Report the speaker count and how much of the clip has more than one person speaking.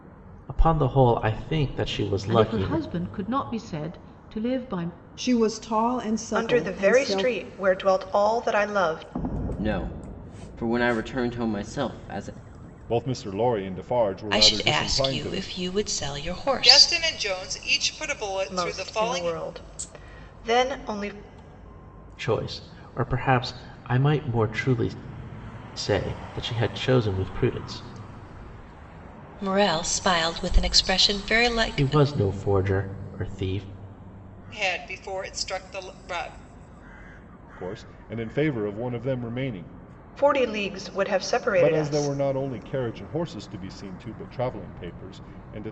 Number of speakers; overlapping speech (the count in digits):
8, about 11%